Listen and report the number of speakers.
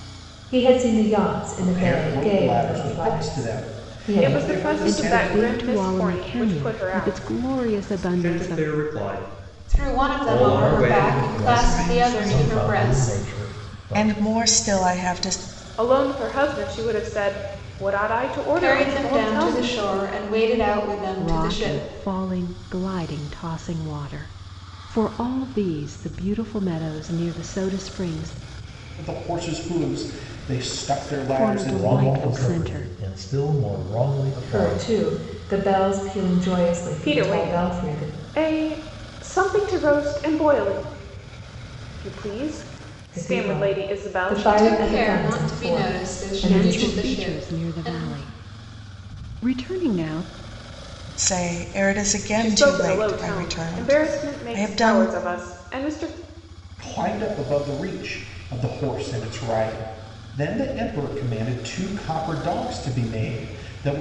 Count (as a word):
eight